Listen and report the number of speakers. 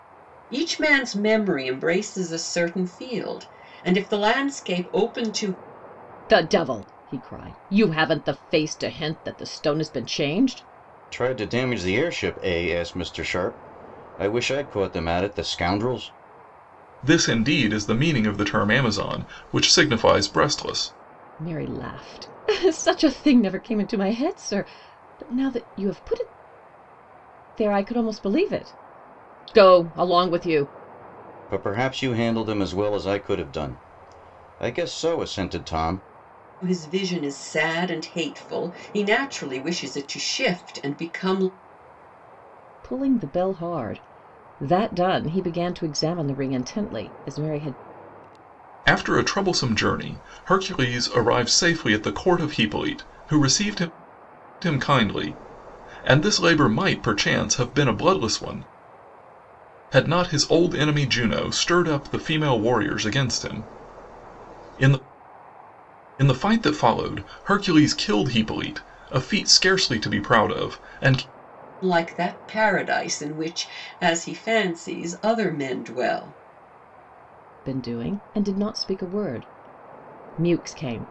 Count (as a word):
four